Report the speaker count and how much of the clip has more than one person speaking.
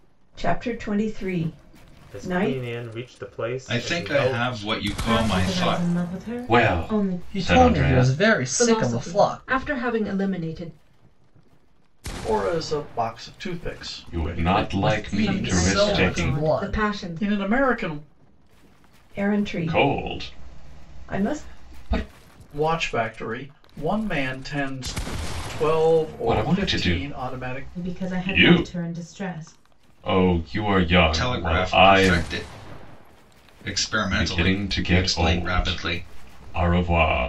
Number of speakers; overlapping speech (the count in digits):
8, about 42%